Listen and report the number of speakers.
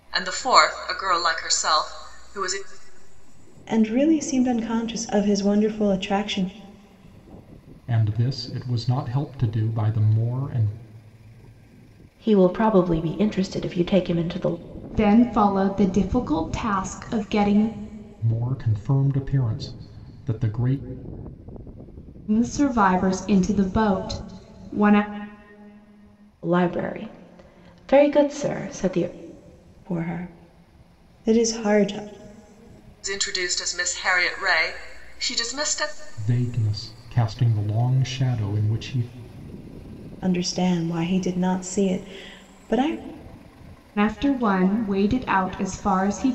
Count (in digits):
5